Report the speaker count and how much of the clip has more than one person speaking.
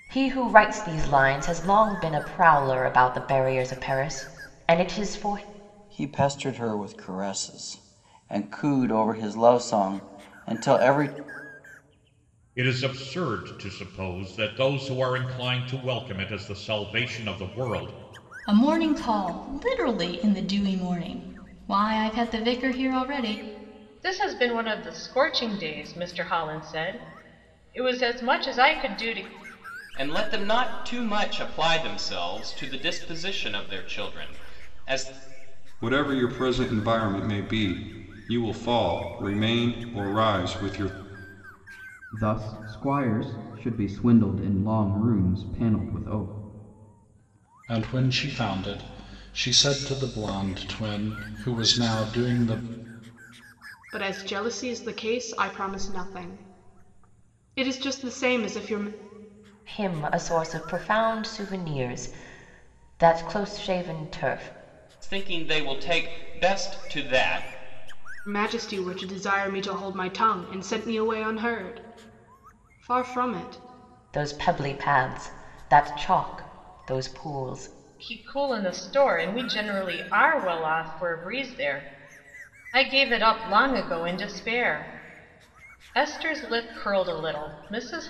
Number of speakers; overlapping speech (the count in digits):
10, no overlap